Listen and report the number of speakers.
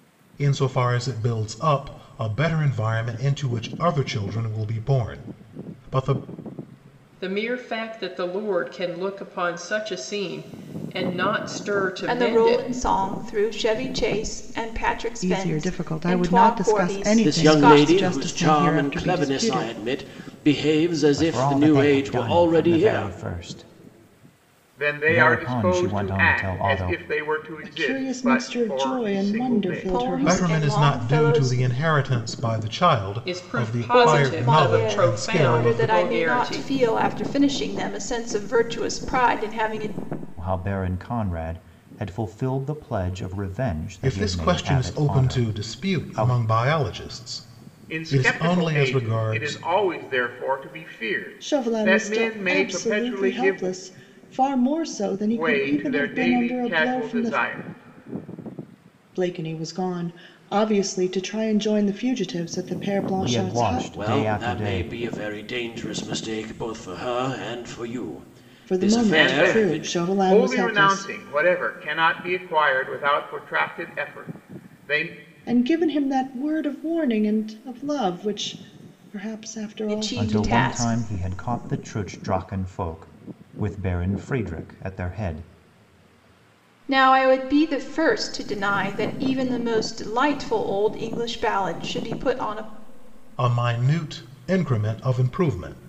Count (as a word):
seven